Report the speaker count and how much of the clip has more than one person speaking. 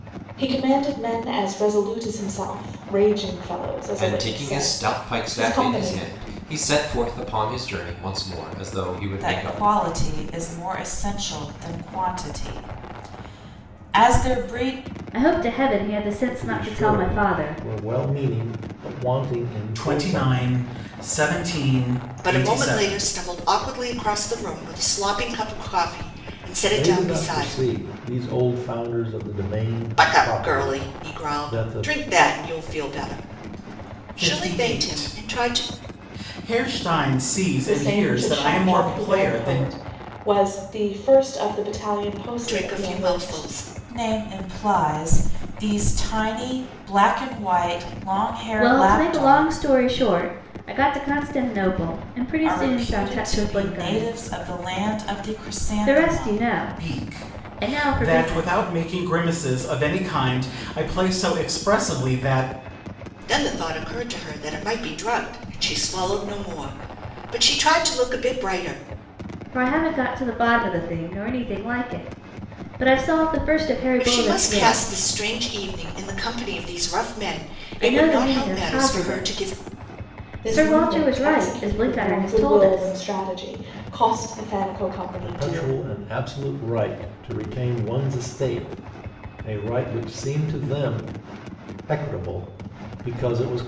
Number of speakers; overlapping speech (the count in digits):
7, about 26%